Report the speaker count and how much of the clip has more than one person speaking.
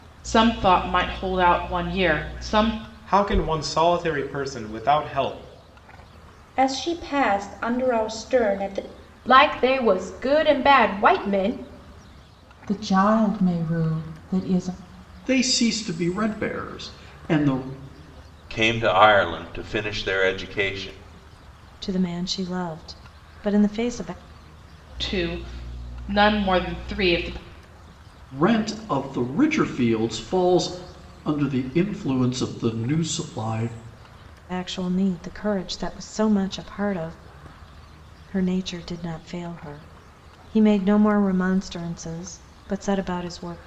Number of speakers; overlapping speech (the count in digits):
8, no overlap